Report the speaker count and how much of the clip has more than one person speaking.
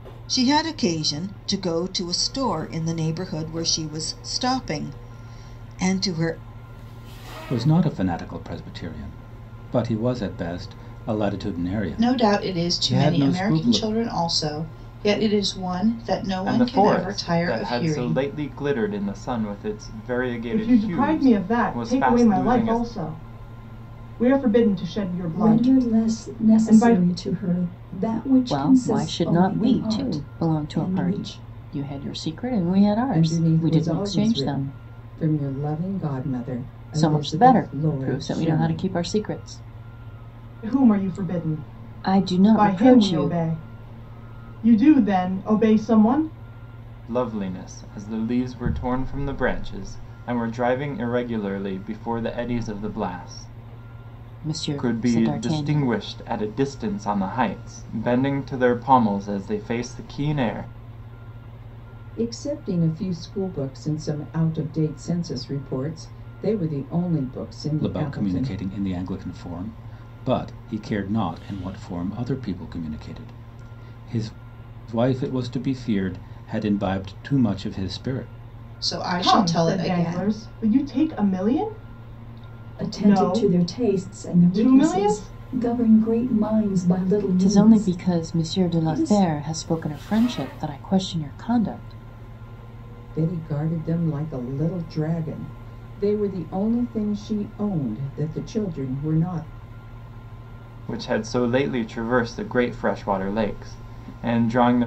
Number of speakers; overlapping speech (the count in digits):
8, about 24%